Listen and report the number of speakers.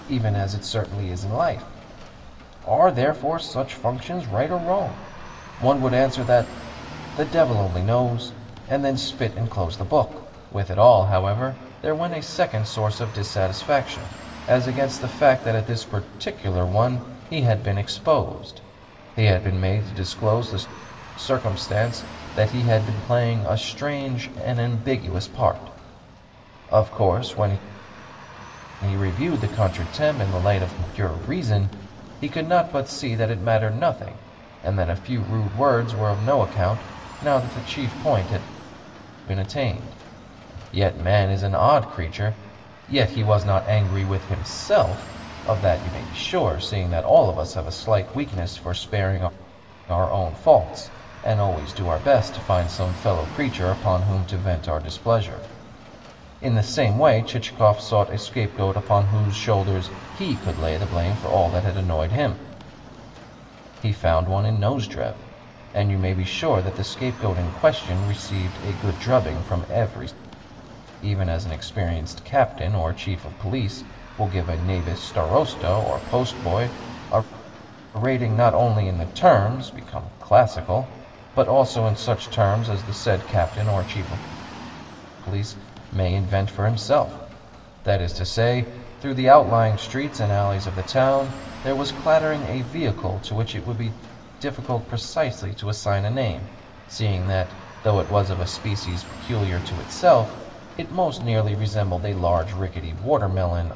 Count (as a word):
one